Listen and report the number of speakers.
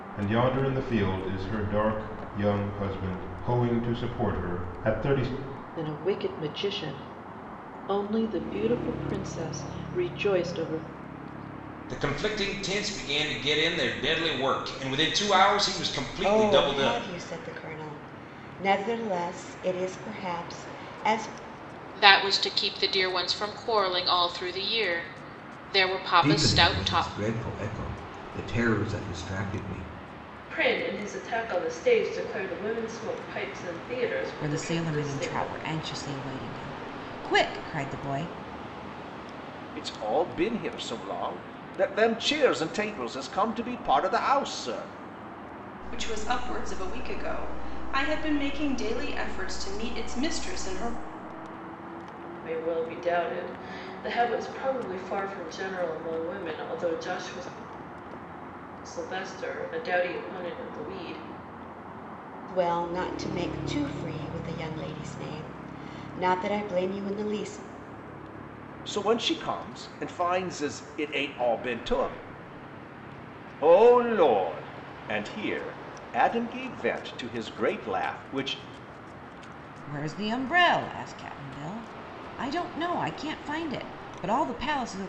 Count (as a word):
ten